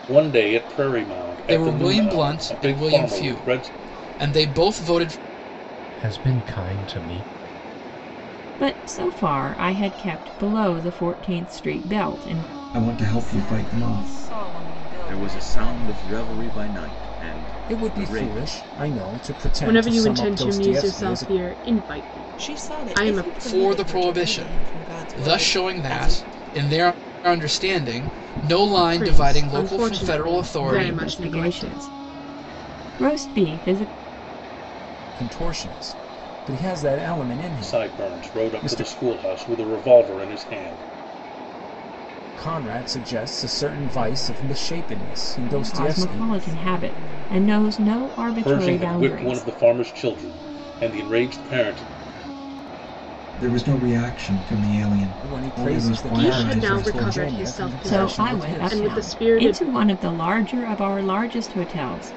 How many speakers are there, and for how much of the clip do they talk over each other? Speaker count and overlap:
10, about 41%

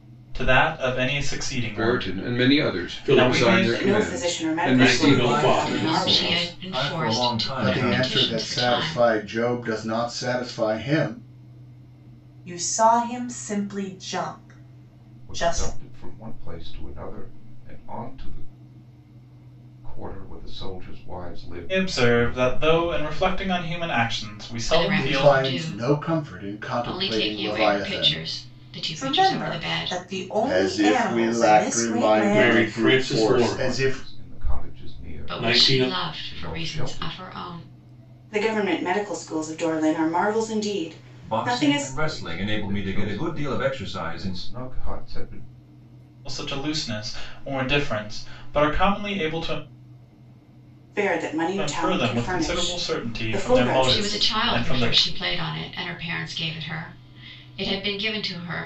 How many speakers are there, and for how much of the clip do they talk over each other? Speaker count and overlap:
9, about 46%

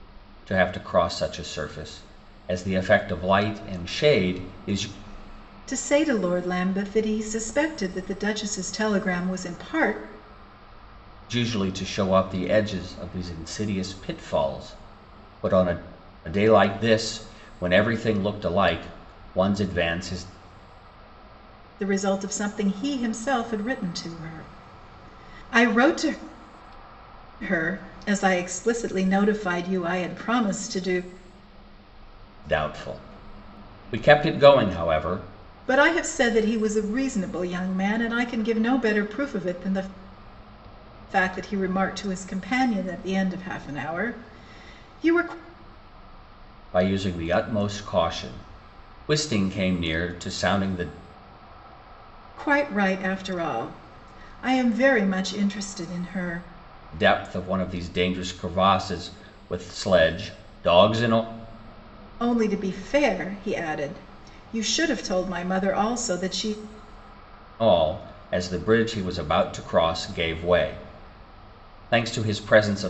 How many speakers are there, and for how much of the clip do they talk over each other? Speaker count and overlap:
2, no overlap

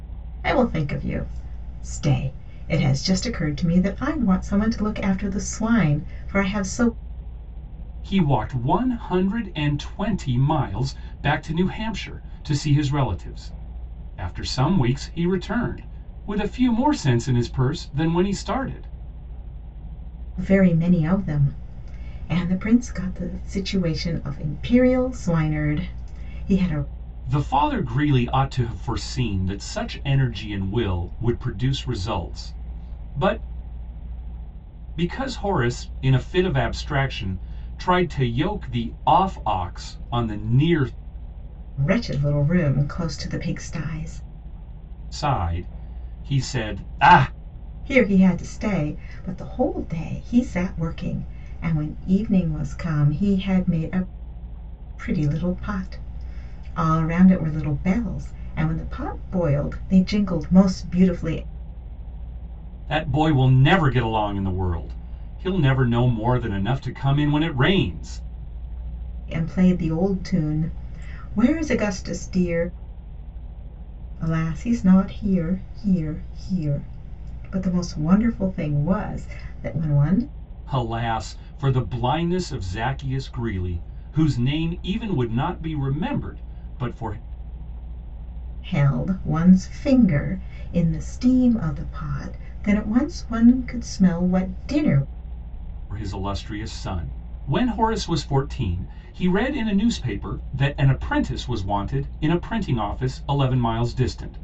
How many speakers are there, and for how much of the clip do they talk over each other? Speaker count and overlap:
2, no overlap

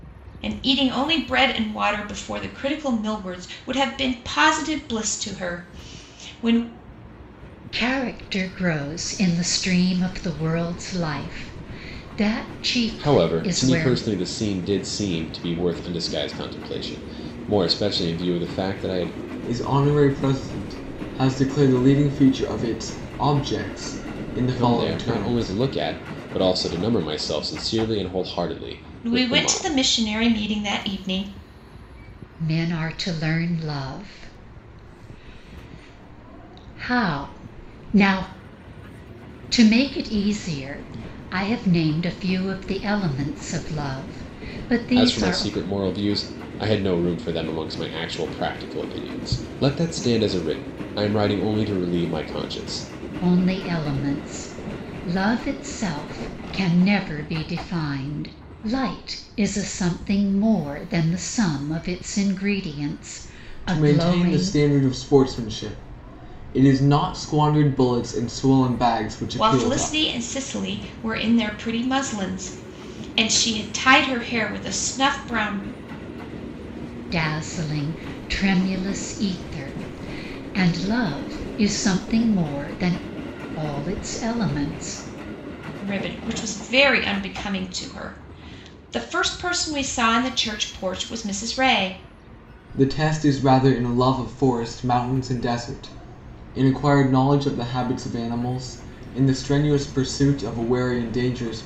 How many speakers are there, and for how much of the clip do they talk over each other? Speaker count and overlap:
4, about 5%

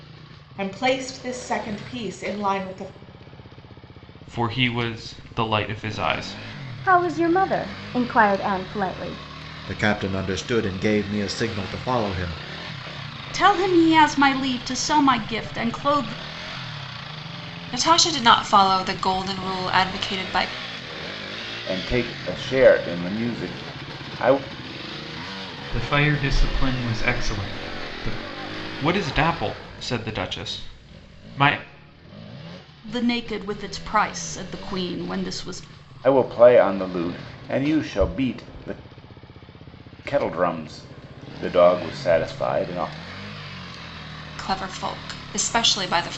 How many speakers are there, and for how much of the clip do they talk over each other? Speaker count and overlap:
8, no overlap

